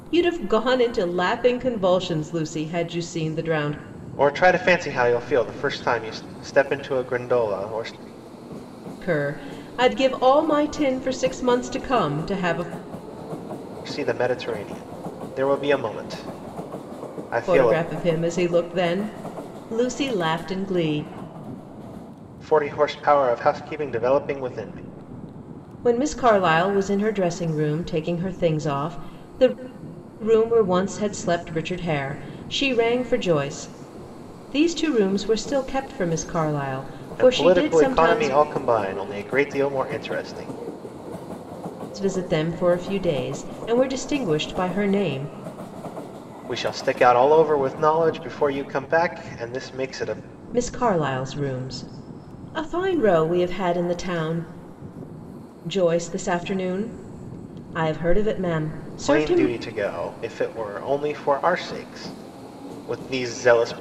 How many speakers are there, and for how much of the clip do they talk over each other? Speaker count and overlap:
2, about 3%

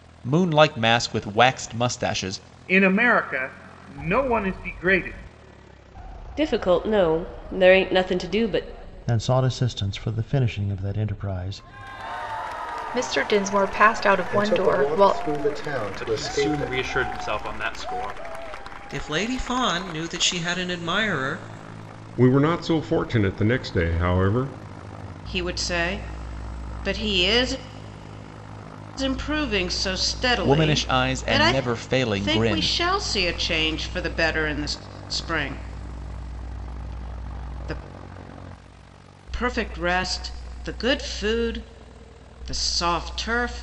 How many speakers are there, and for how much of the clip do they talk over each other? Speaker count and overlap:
10, about 9%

